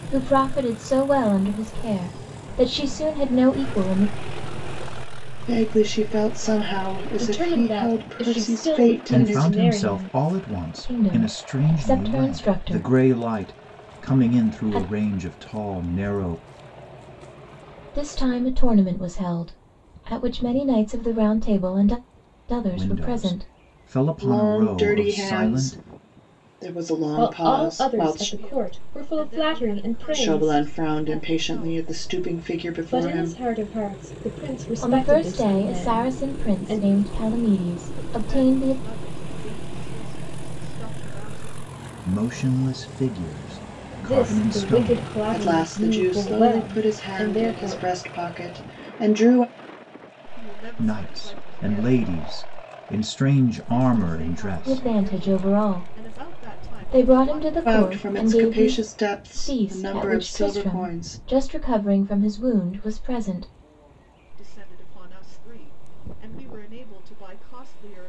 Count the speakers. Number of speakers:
five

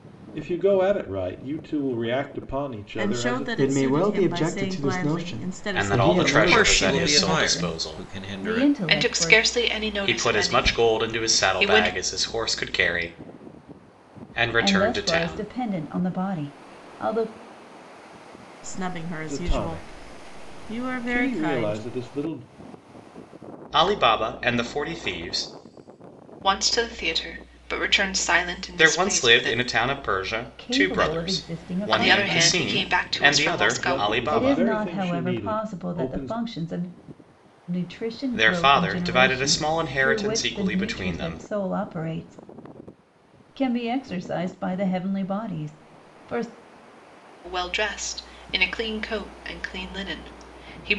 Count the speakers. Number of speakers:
seven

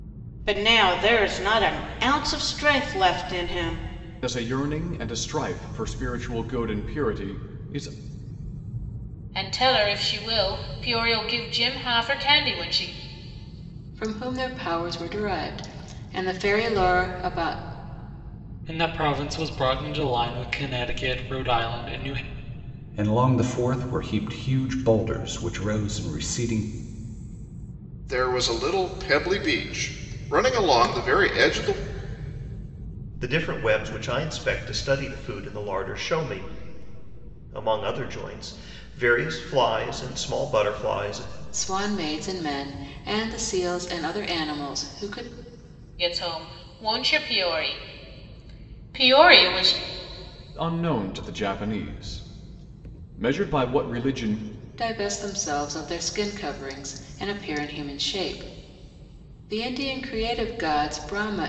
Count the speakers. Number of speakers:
eight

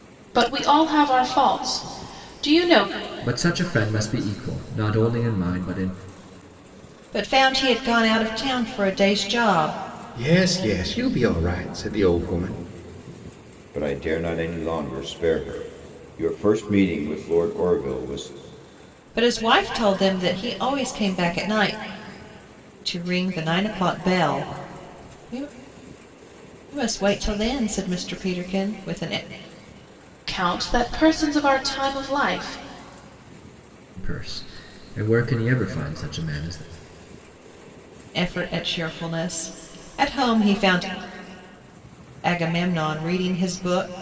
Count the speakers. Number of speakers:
five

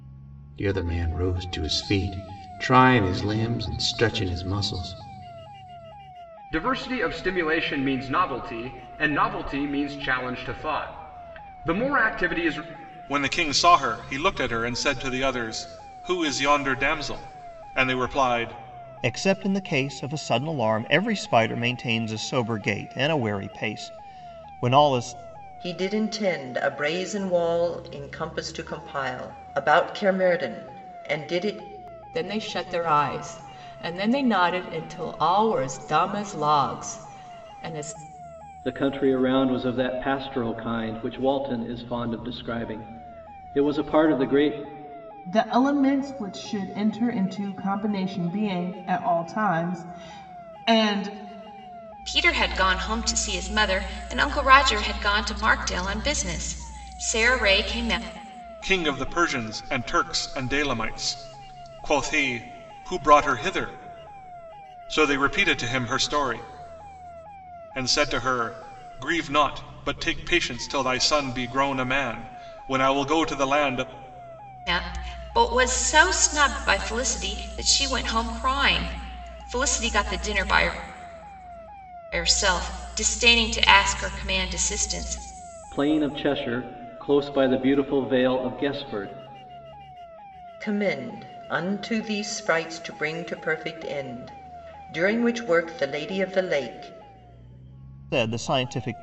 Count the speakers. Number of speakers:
nine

